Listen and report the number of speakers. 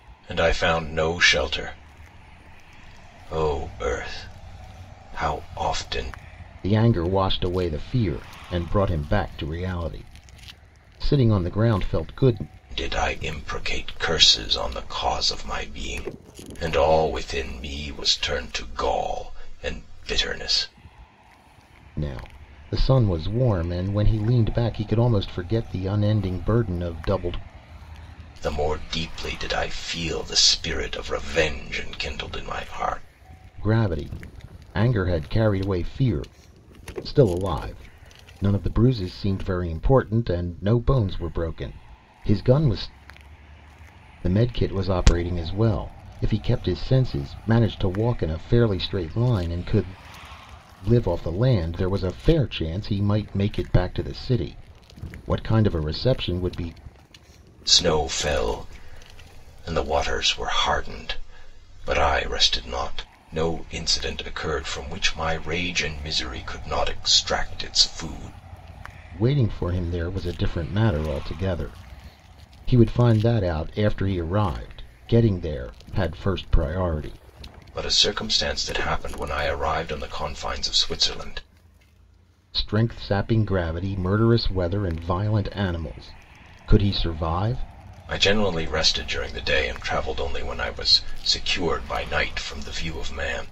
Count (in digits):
2